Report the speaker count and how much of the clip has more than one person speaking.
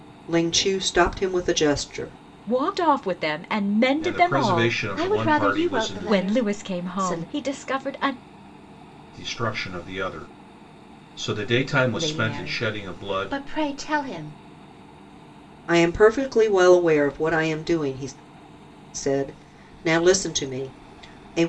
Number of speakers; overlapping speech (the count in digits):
4, about 21%